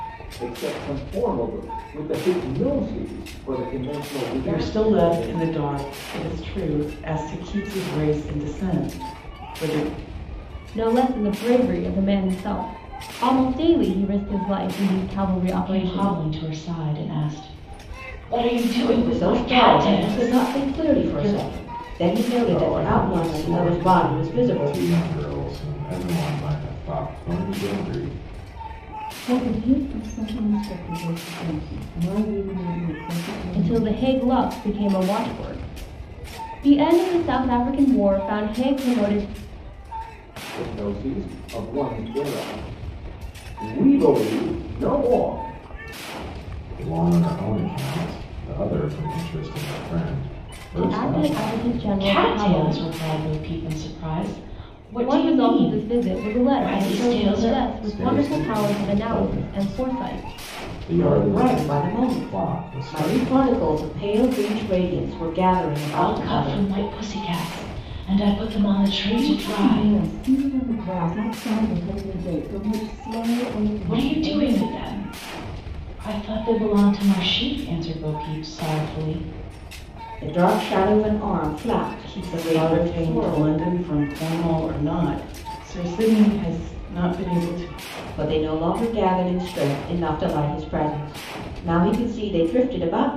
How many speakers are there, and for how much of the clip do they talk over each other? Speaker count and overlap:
seven, about 22%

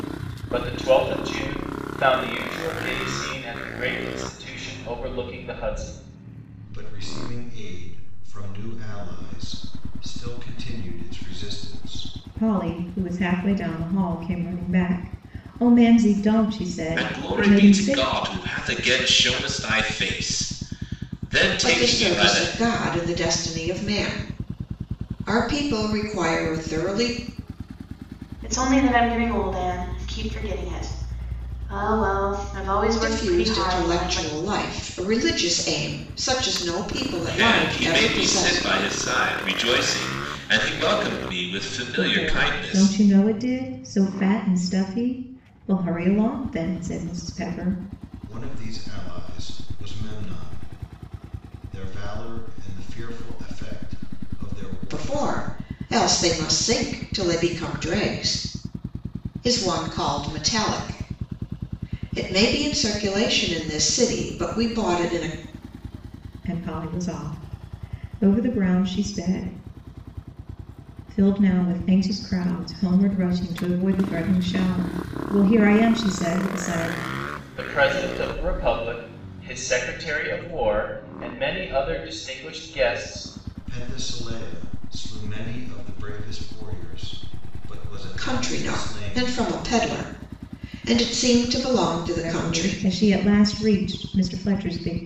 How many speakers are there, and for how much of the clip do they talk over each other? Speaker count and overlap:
six, about 9%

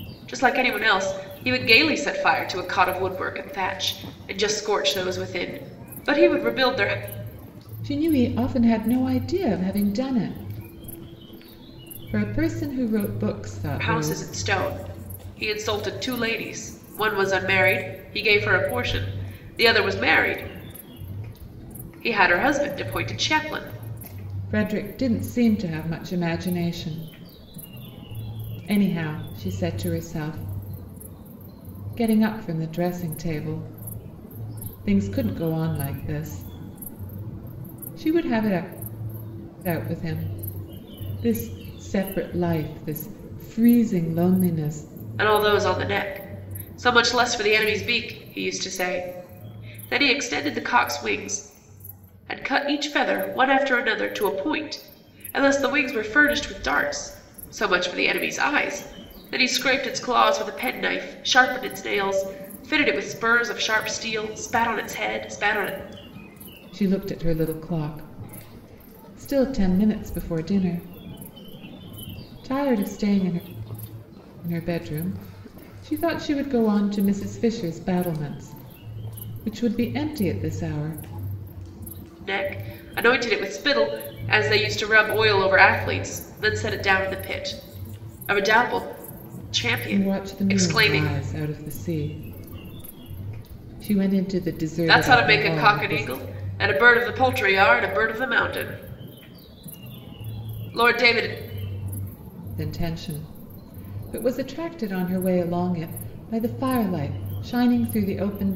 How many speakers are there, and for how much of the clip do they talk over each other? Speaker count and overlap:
two, about 3%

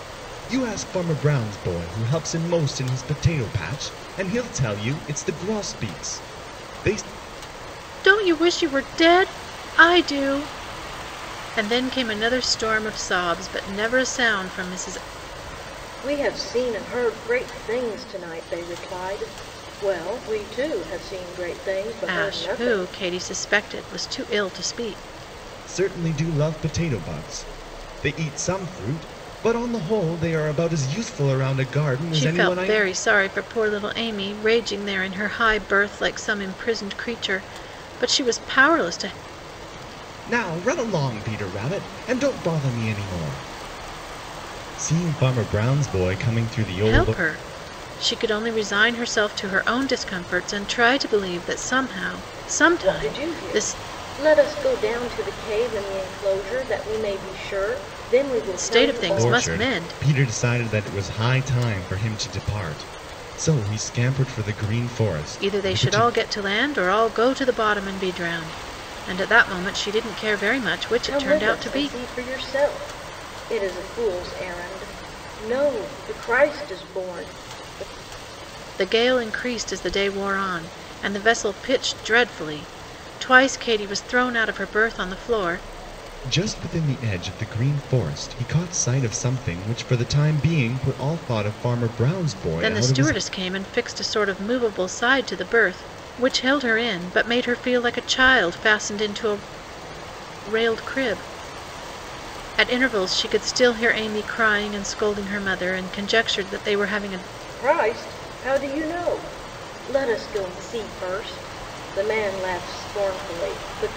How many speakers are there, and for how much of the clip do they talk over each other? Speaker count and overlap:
three, about 6%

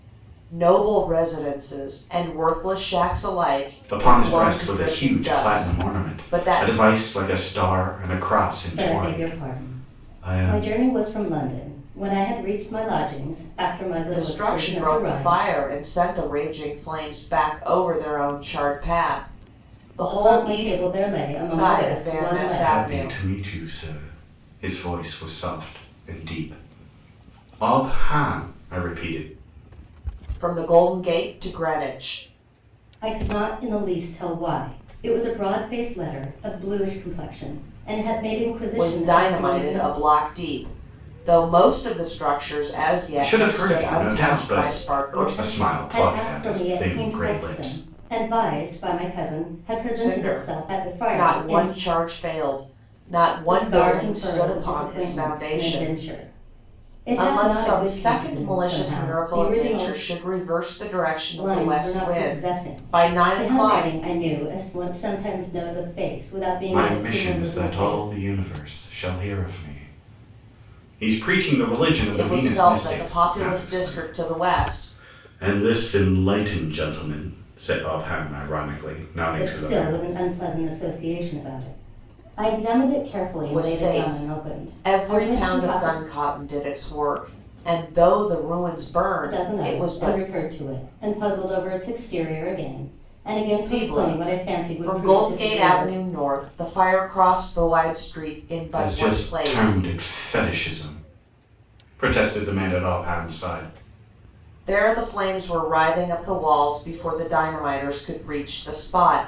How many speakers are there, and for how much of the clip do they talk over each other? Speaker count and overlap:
three, about 33%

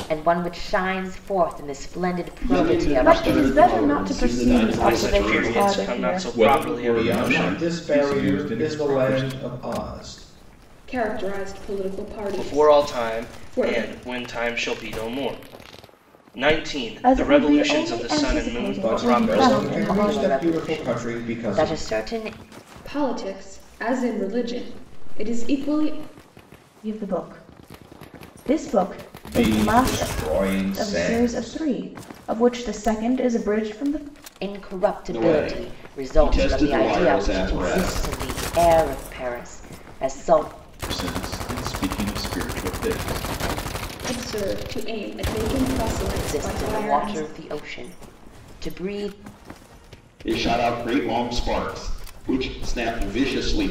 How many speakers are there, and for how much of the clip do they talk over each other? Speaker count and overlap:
seven, about 35%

